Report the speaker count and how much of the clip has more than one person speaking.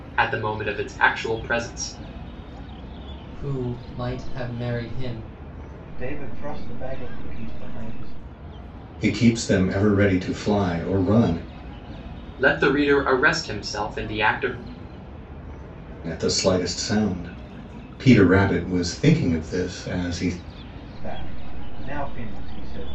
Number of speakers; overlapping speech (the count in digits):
4, no overlap